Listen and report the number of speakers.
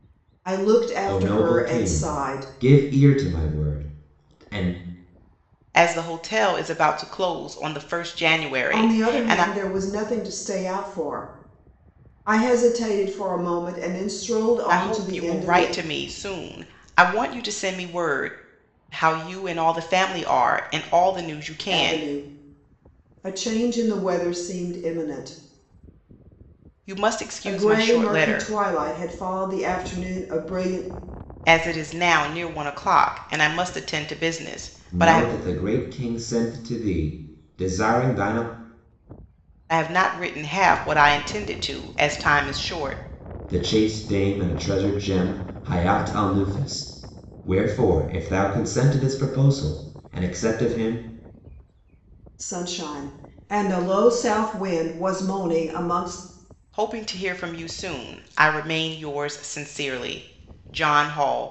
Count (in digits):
3